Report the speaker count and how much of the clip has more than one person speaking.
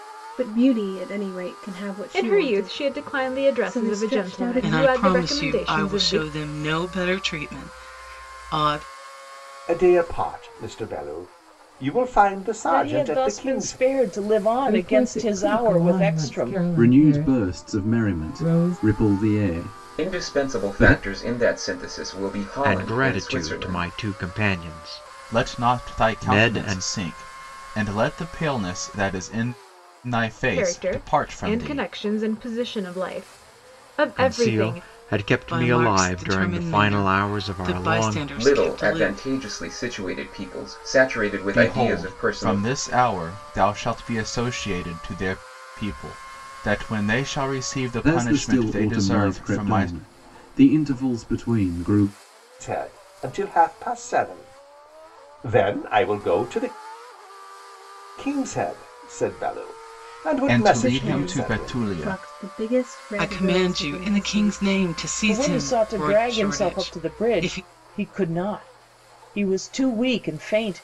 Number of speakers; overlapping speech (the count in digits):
10, about 40%